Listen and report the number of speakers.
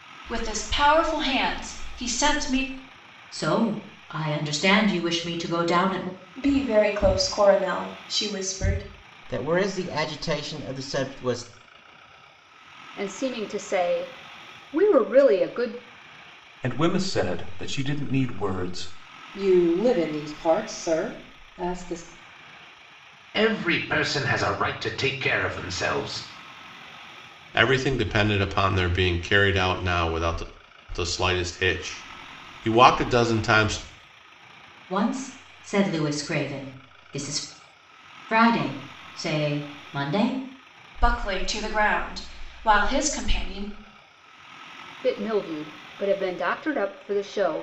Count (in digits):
9